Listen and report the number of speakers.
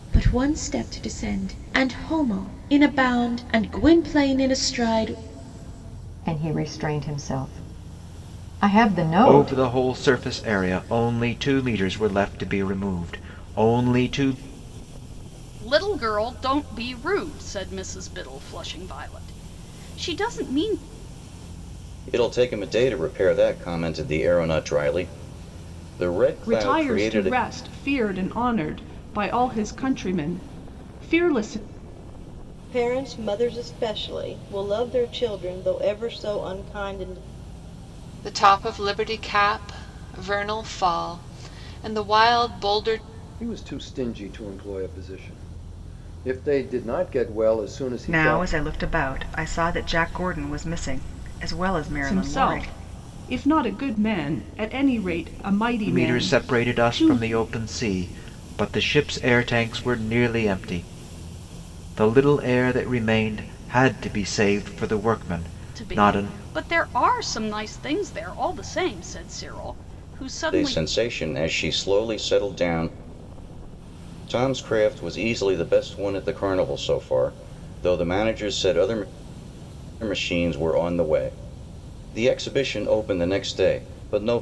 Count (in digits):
10